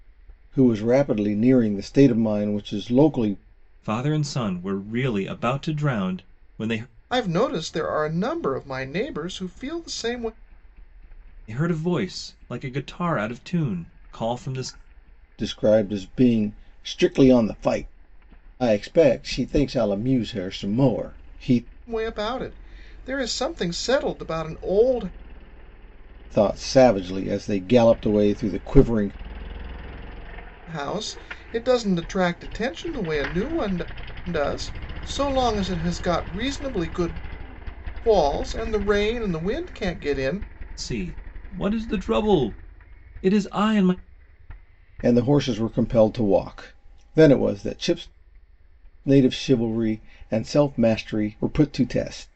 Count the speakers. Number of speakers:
three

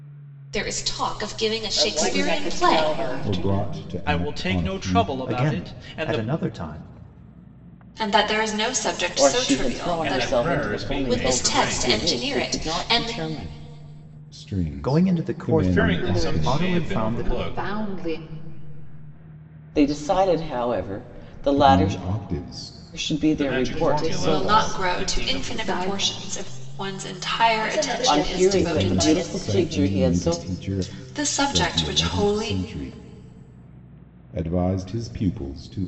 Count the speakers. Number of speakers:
nine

